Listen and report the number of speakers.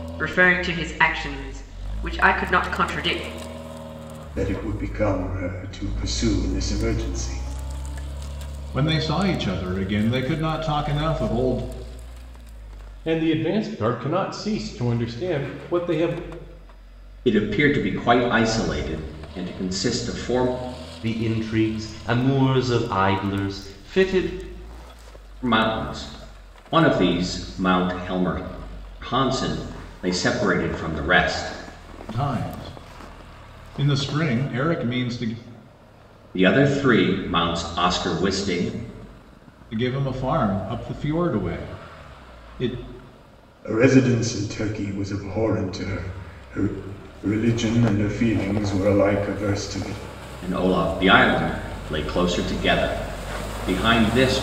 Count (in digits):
6